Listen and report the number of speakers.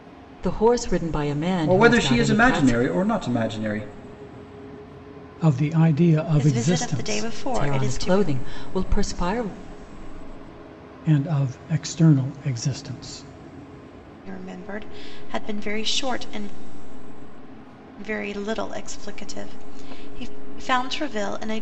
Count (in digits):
4